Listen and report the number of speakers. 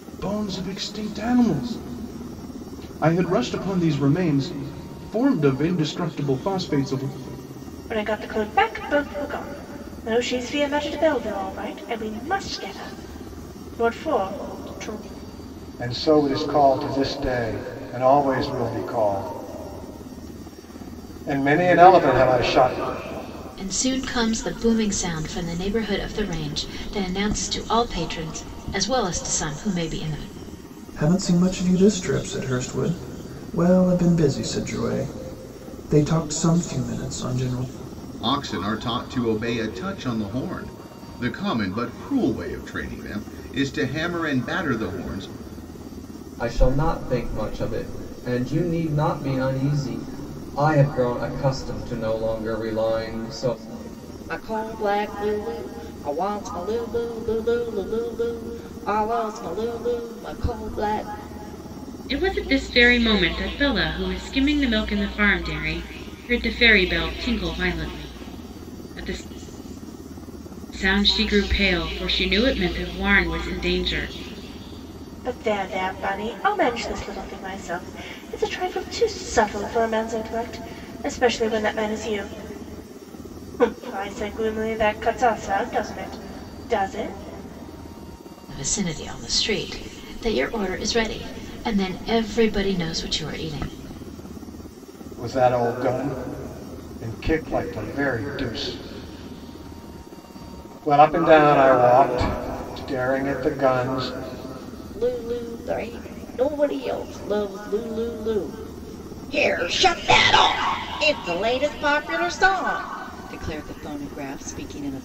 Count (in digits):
9